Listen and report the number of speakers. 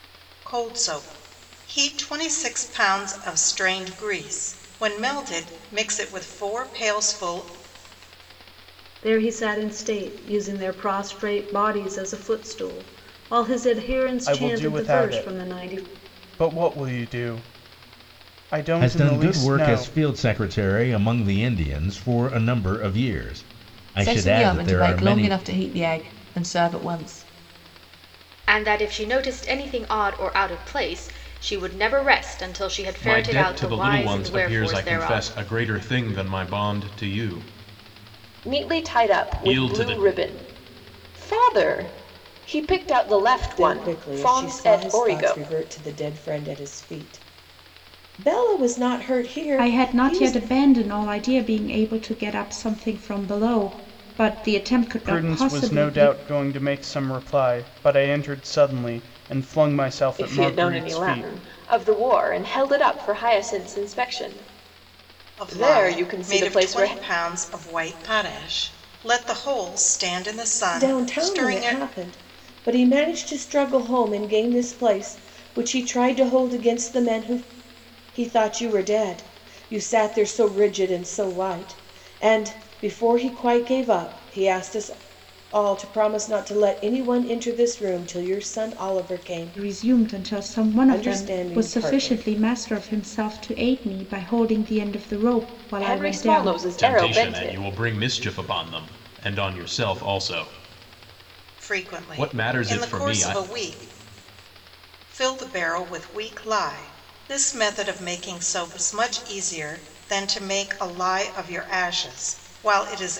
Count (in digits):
10